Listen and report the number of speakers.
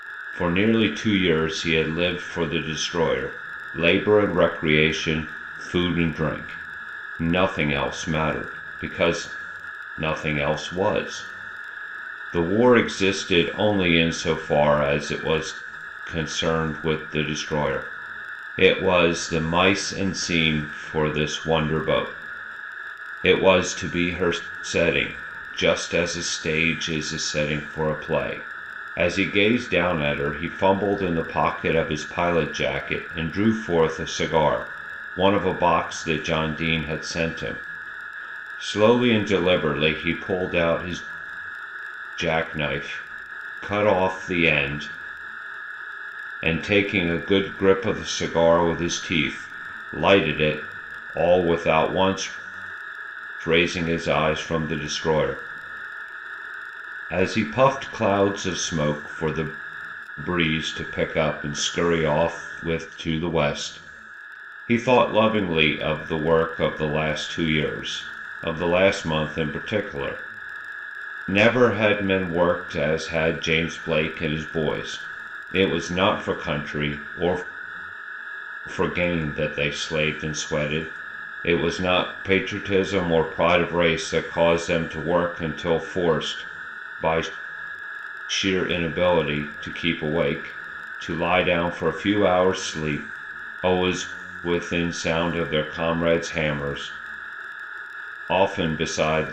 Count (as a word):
one